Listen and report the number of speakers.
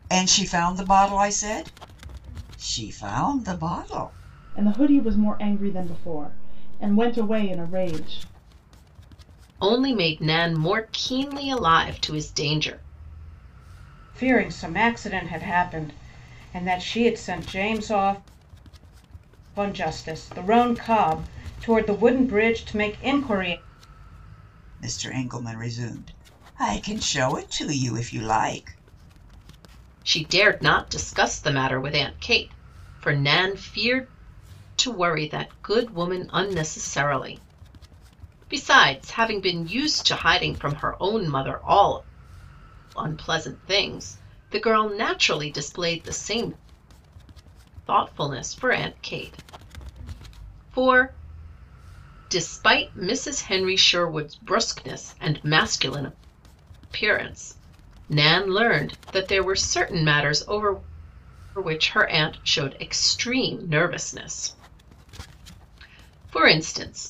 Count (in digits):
4